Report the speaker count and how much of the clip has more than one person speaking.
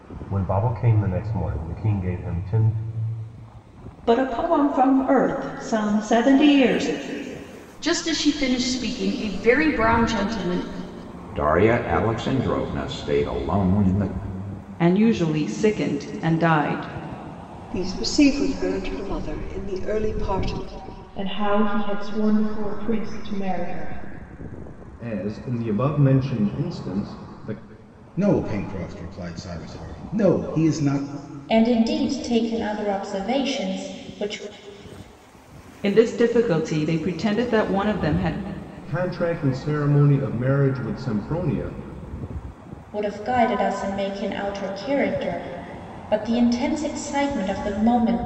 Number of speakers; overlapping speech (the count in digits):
10, no overlap